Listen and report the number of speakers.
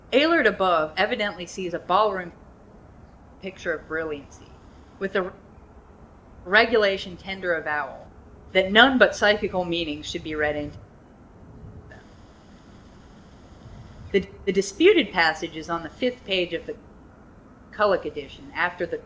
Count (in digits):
1